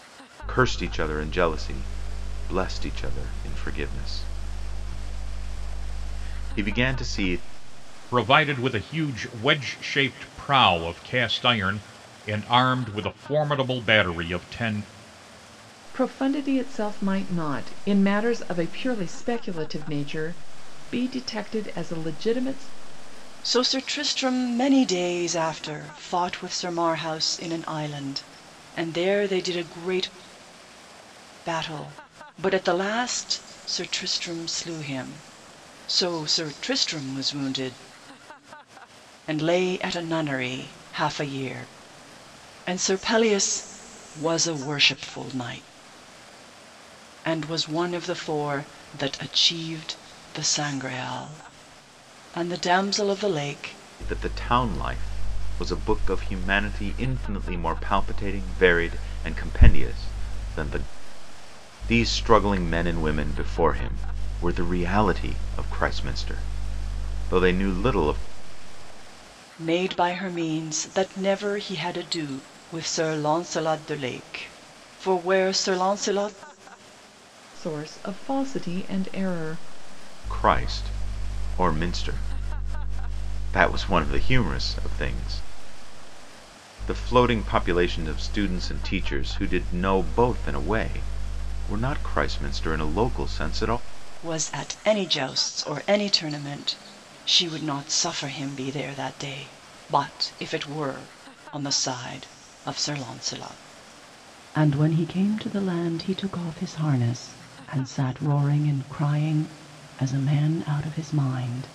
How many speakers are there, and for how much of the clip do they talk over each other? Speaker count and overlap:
four, no overlap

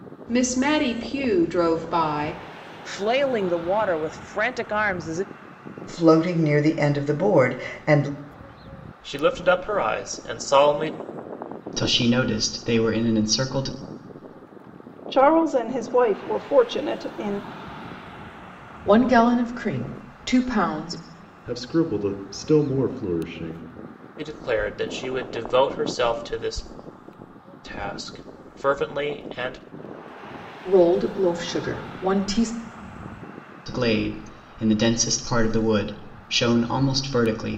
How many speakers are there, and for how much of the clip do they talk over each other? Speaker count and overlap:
eight, no overlap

